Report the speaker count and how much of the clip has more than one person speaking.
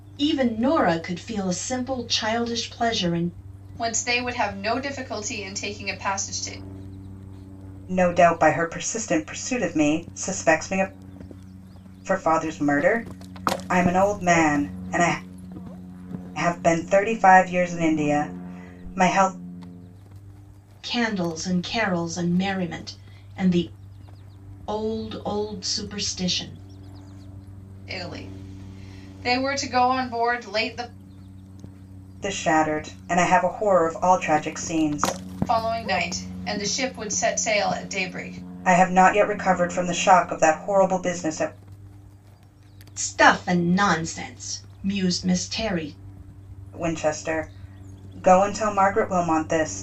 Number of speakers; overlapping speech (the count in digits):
3, no overlap